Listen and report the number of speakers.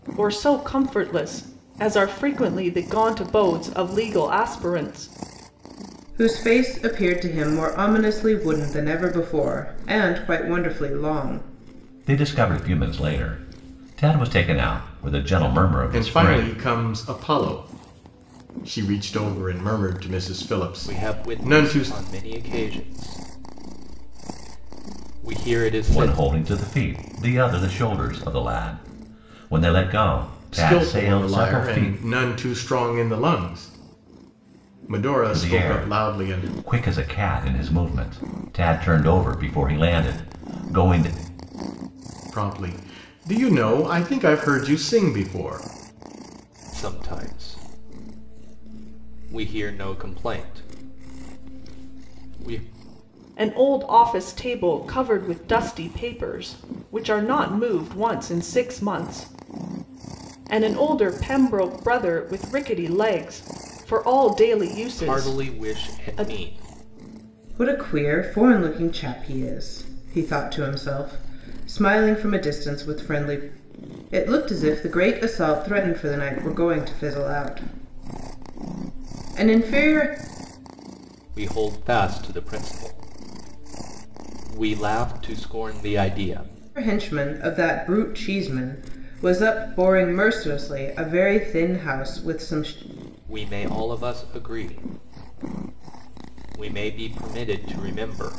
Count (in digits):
5